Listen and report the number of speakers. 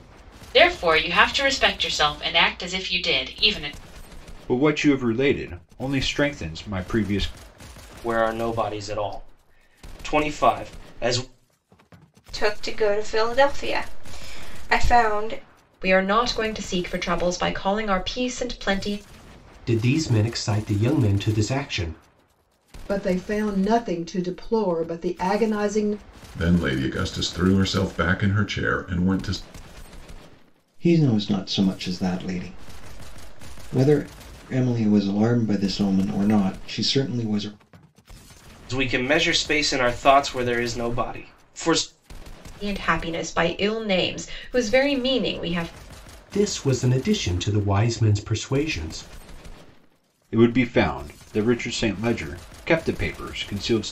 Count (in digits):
9